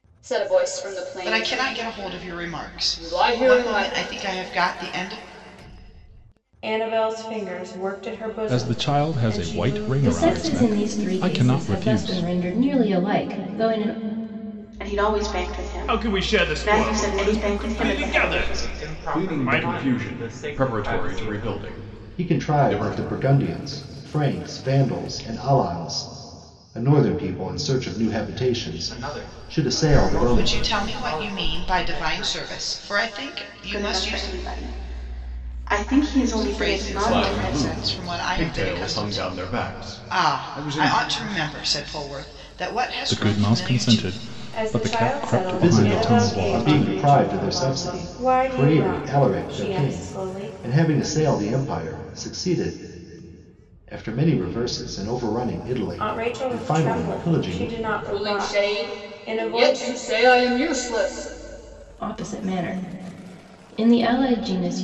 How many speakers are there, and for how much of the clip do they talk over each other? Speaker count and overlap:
10, about 50%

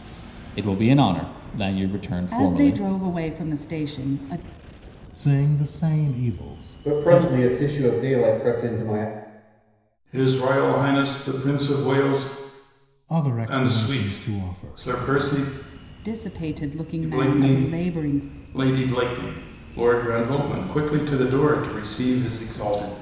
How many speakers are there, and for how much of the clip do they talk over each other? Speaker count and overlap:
5, about 16%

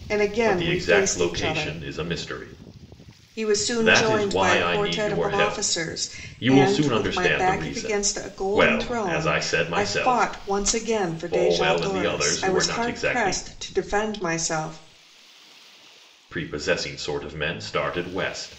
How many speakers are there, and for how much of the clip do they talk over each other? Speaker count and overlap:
2, about 48%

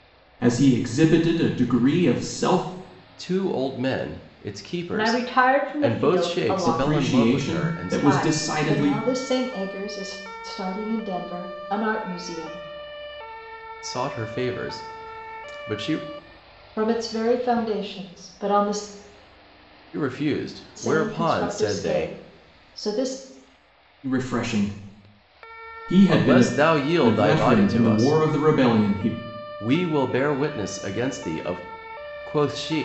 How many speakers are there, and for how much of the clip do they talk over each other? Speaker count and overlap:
3, about 20%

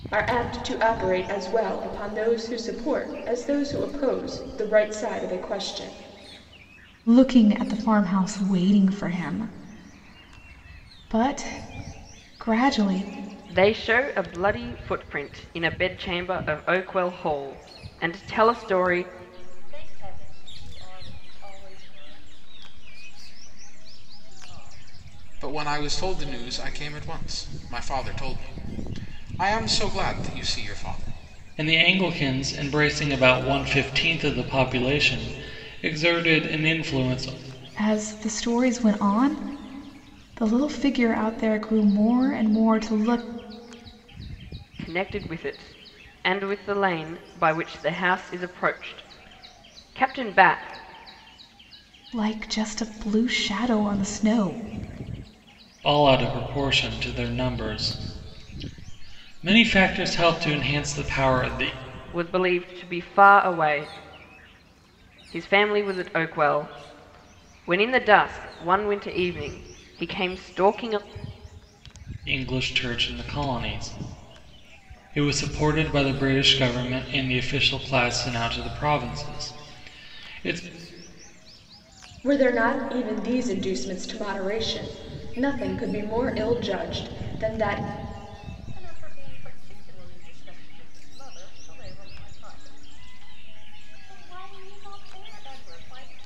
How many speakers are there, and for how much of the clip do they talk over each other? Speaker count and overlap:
6, no overlap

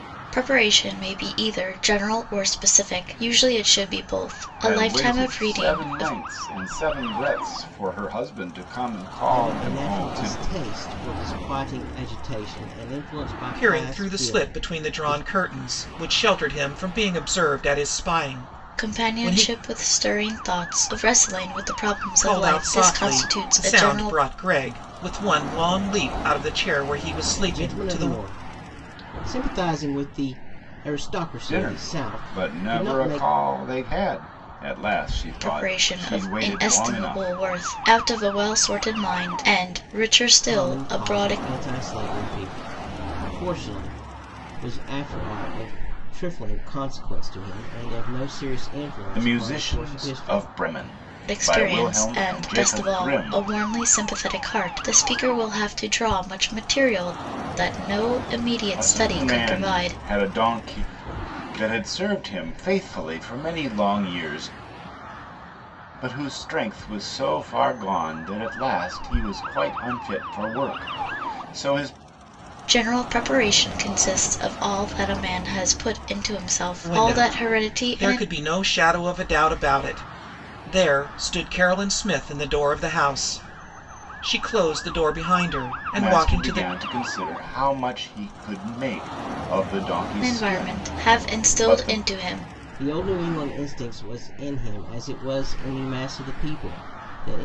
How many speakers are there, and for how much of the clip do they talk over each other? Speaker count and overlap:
4, about 22%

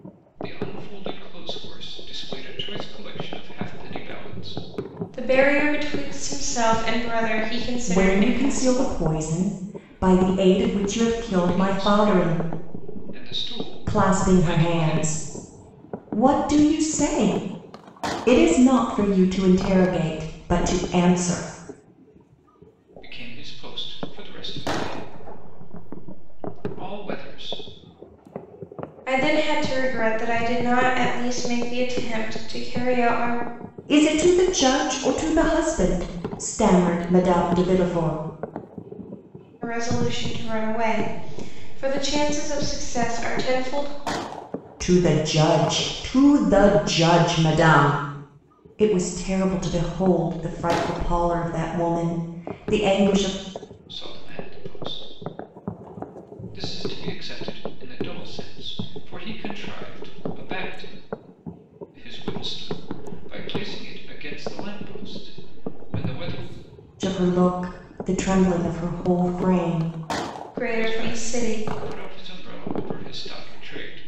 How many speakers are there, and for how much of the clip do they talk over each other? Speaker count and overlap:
3, about 6%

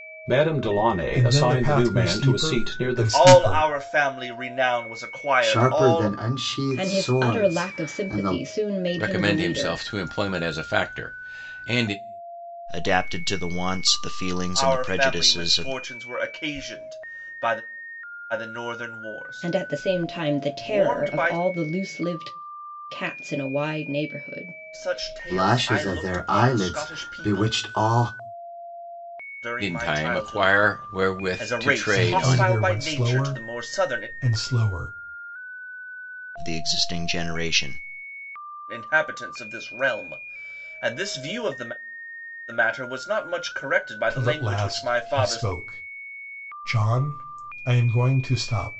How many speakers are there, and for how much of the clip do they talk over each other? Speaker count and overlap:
7, about 35%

